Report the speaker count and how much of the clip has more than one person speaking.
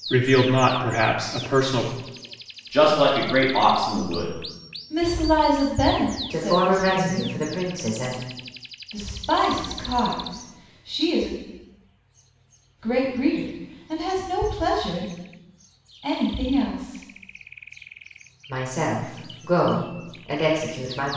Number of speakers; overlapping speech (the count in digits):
4, about 5%